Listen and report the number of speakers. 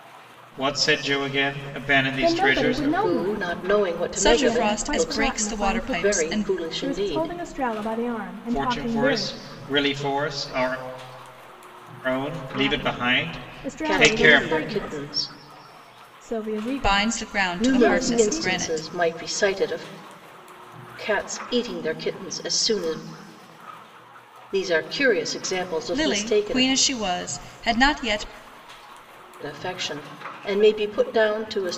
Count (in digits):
4